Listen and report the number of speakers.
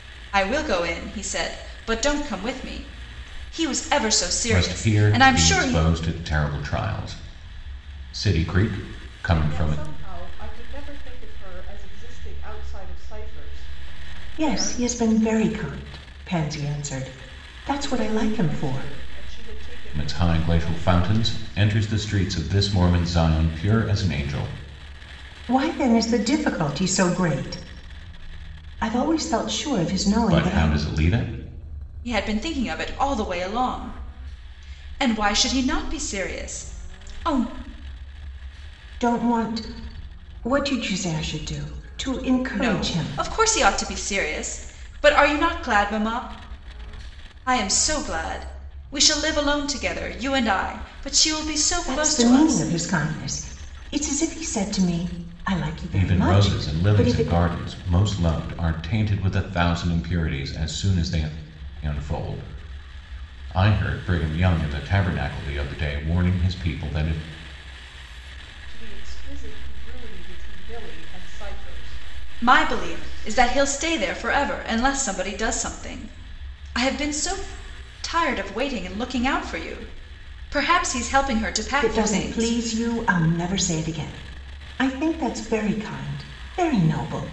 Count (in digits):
4